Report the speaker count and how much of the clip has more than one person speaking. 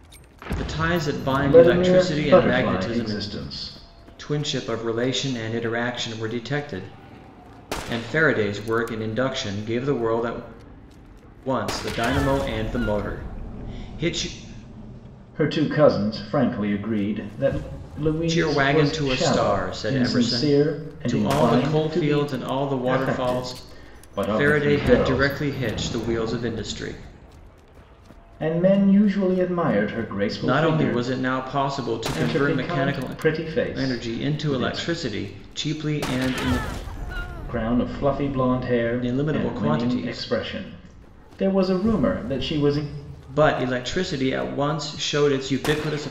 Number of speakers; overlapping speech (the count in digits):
2, about 24%